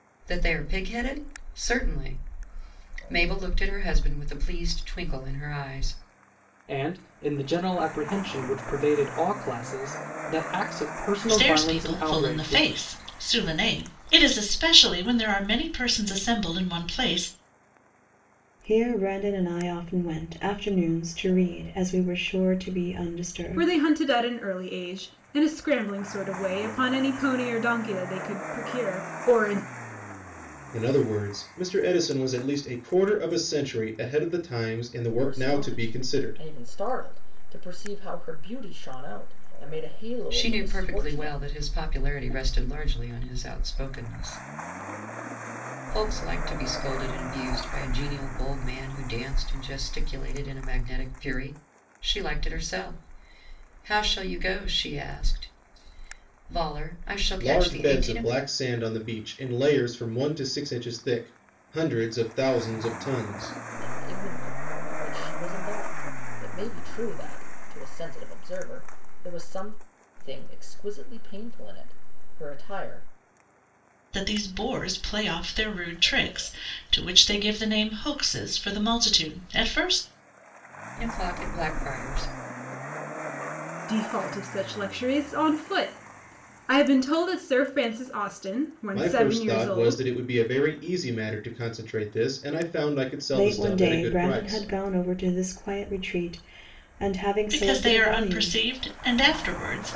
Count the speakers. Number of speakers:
seven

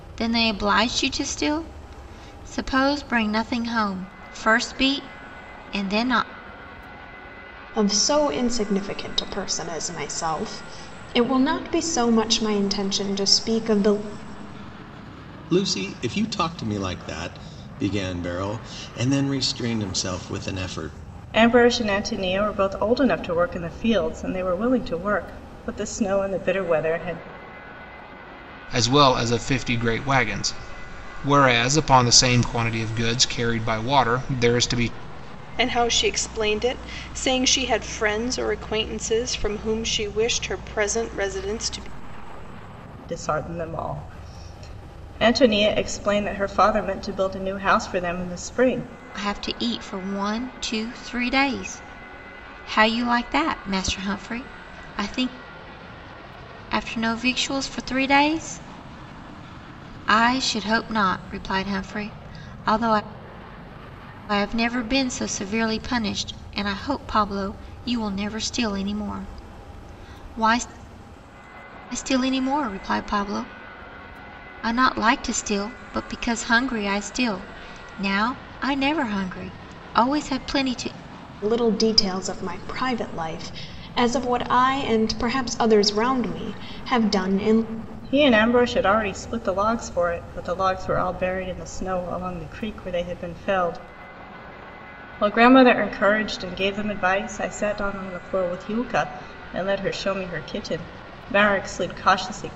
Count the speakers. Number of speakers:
six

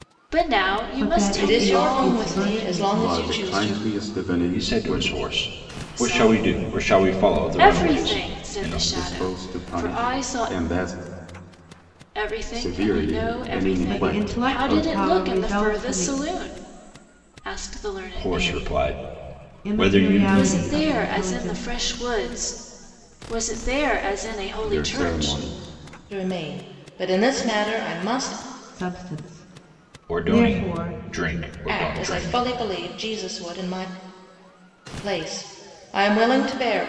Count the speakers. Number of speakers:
five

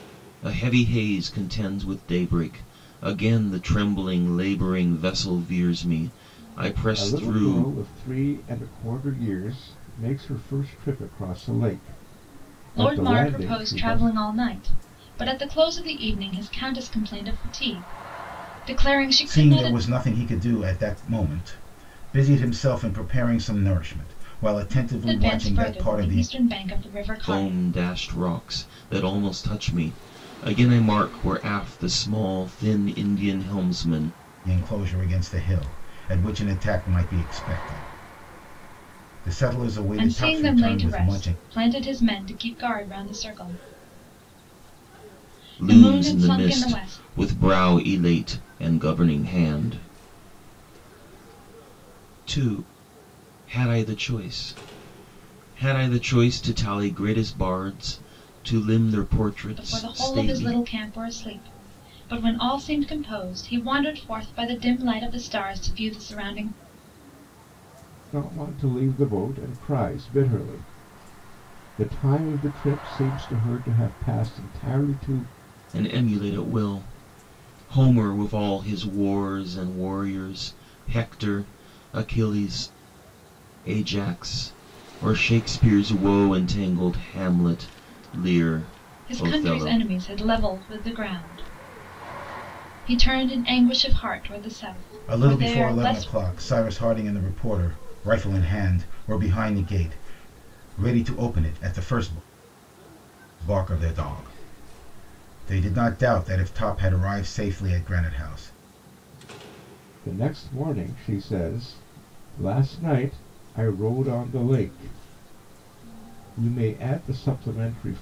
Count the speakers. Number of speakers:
four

